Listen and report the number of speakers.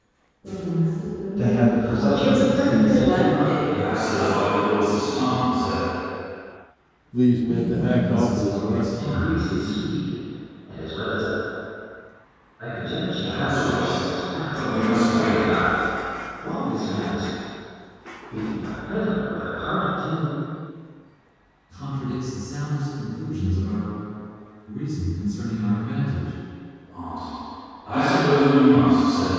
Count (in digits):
7